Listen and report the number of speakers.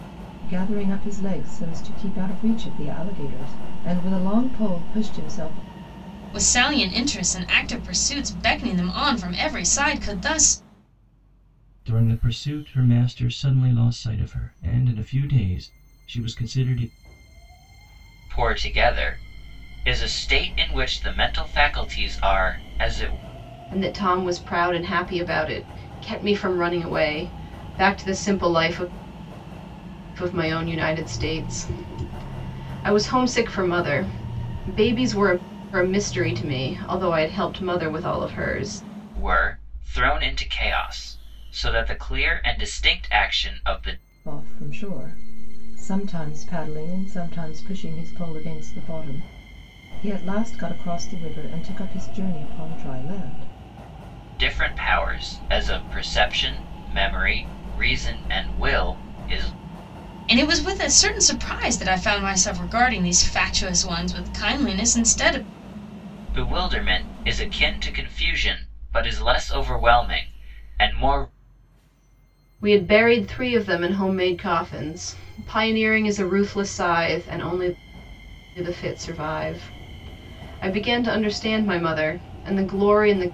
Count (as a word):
five